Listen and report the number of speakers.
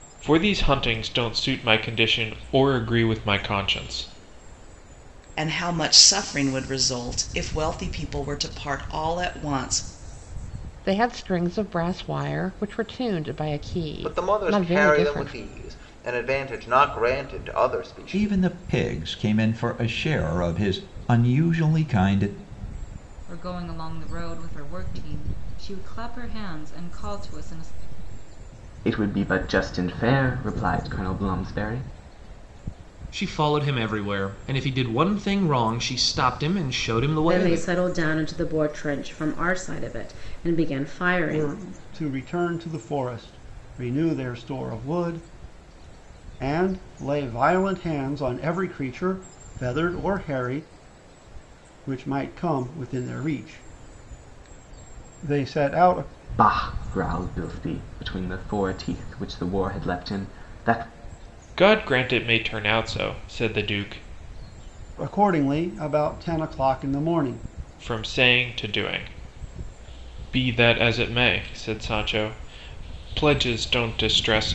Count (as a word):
ten